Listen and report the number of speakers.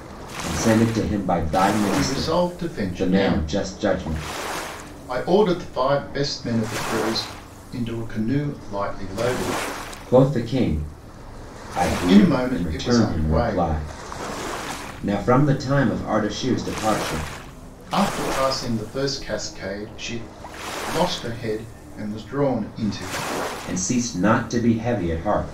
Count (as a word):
two